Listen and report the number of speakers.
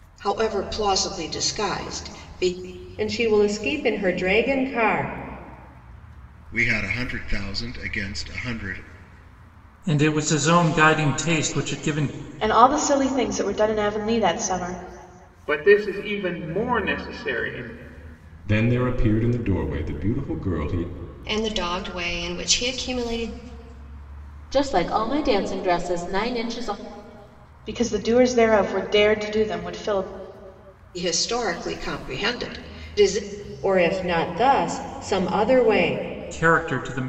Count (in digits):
9